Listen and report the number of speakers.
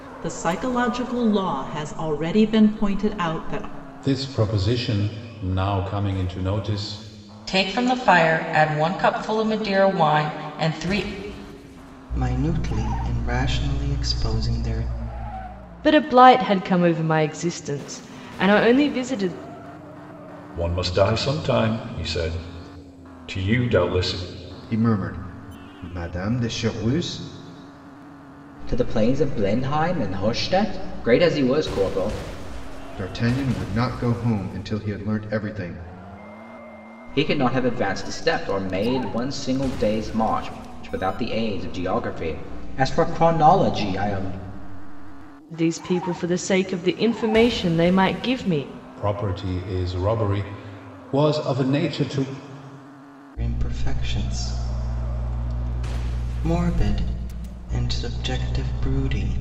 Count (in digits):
8